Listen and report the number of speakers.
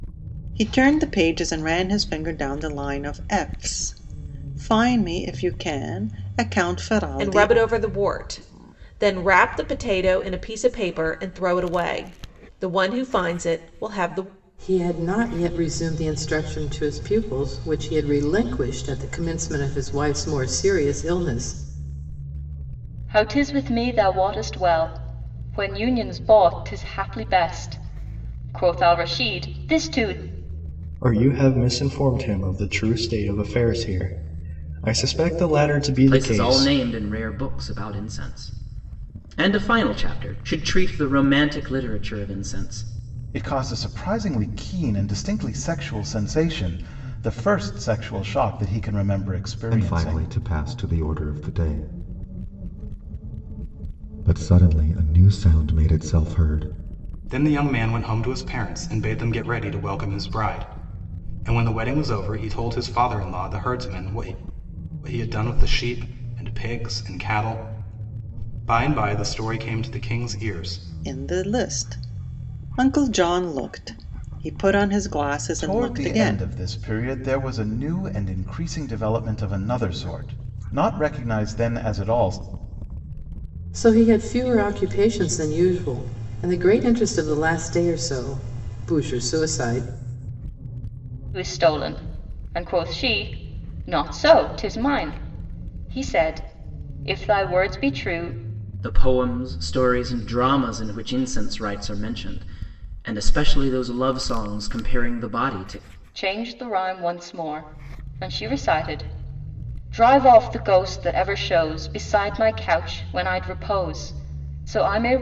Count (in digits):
9